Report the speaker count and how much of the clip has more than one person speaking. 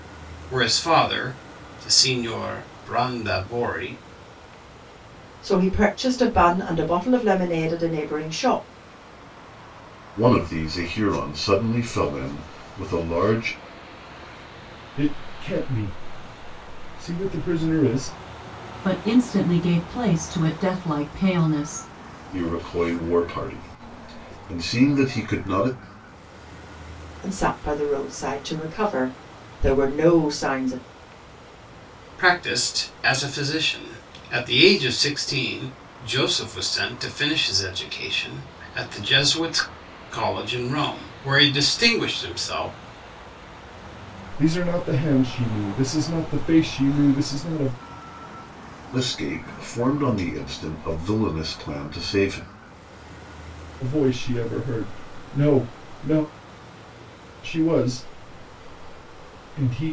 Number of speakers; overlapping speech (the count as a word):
five, no overlap